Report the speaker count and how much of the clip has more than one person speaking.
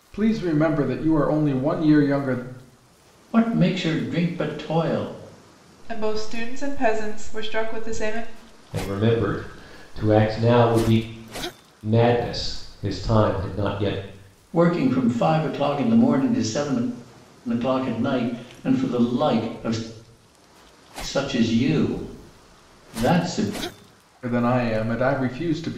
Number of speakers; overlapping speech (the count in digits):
4, no overlap